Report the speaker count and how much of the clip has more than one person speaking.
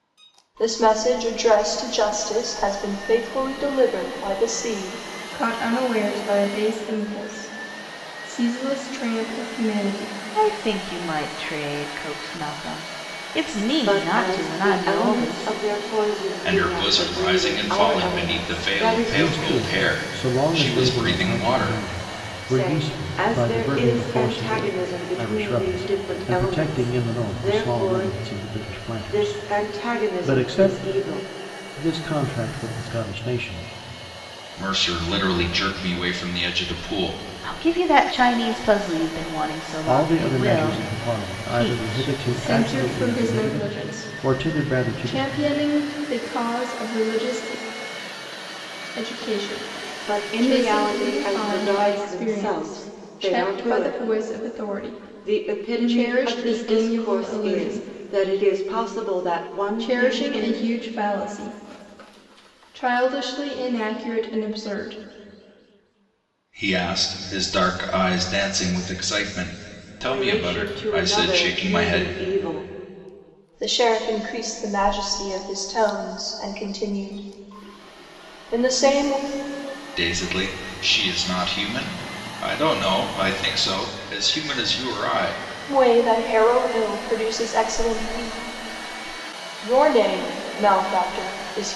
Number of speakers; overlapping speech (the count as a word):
six, about 33%